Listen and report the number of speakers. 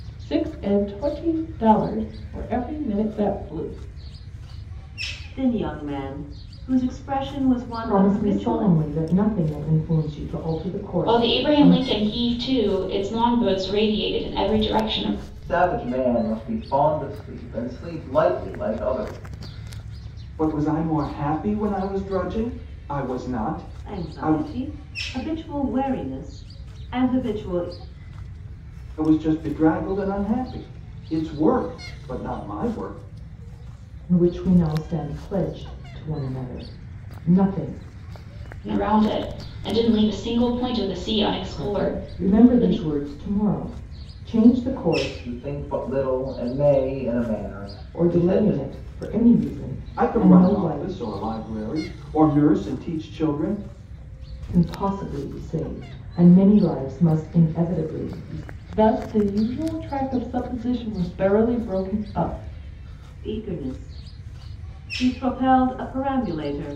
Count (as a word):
six